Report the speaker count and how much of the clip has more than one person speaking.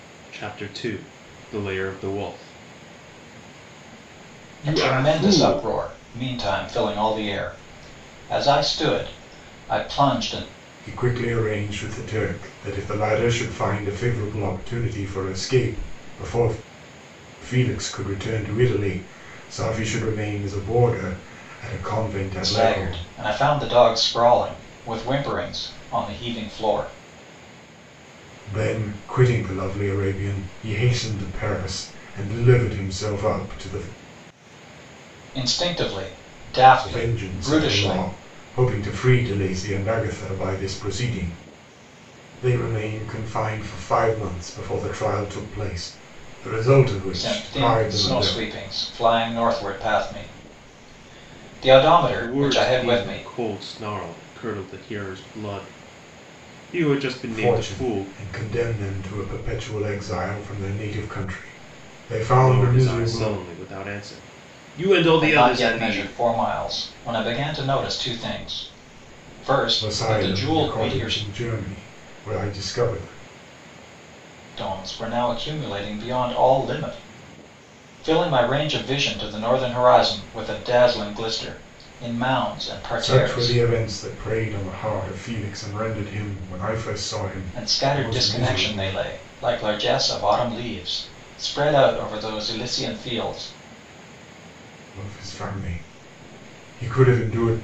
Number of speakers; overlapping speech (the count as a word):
three, about 12%